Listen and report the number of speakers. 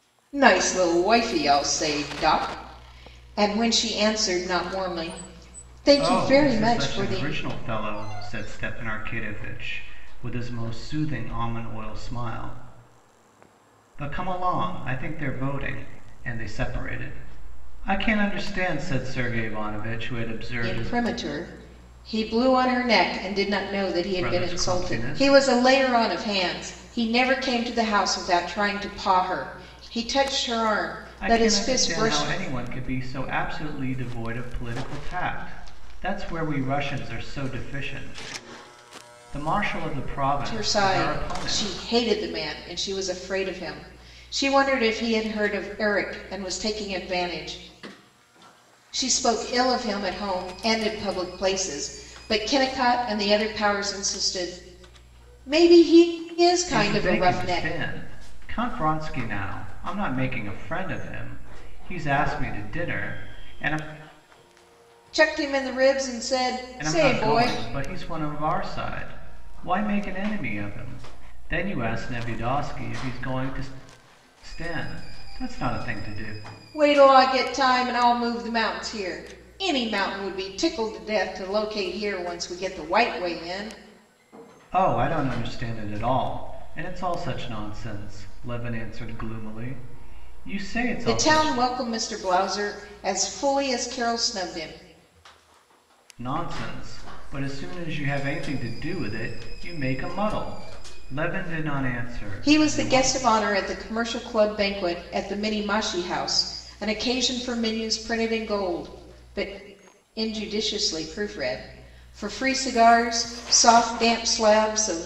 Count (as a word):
two